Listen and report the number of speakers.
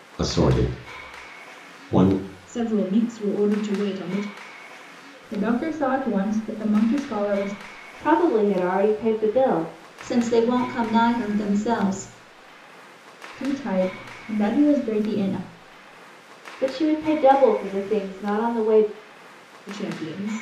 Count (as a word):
five